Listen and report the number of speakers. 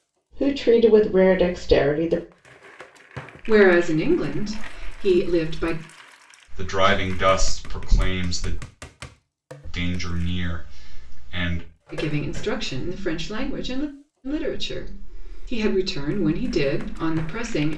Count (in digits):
3